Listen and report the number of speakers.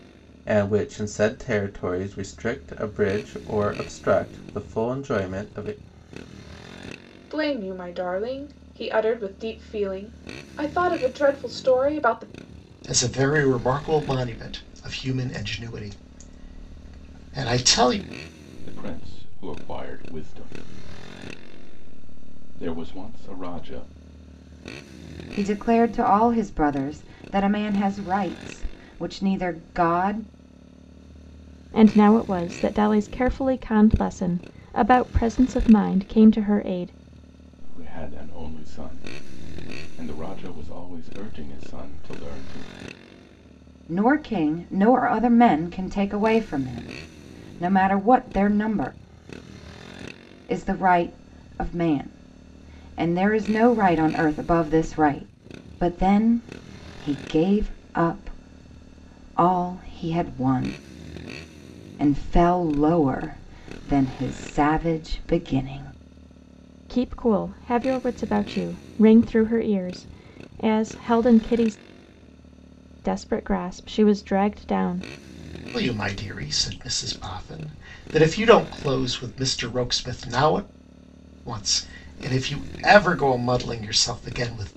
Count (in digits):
6